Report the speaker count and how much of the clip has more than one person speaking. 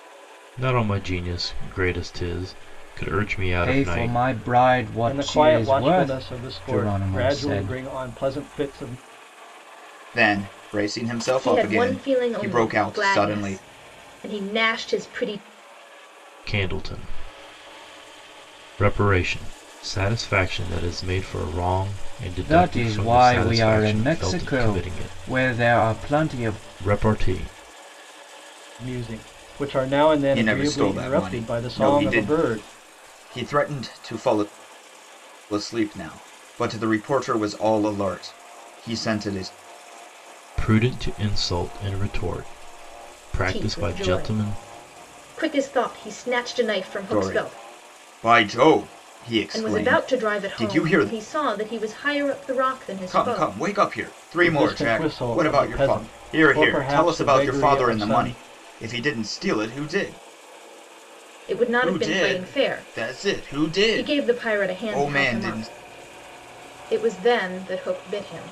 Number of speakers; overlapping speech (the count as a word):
five, about 34%